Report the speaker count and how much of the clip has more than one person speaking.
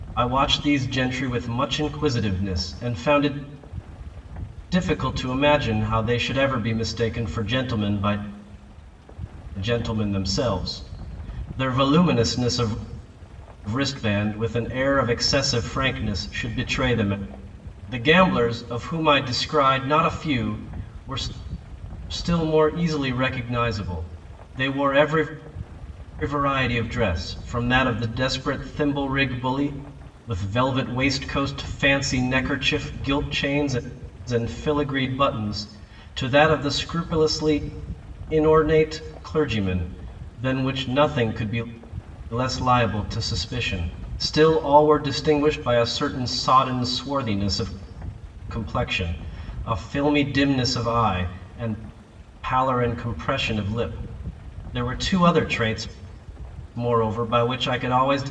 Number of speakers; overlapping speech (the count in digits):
1, no overlap